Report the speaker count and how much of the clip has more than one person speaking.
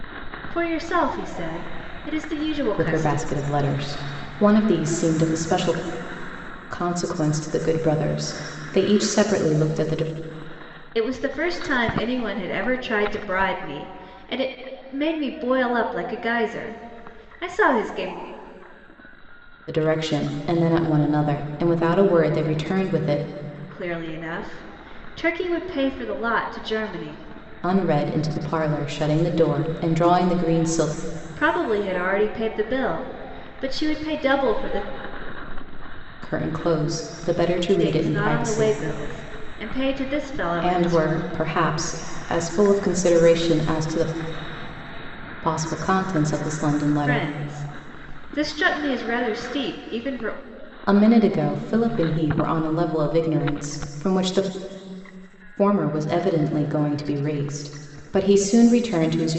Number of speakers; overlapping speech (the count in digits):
2, about 4%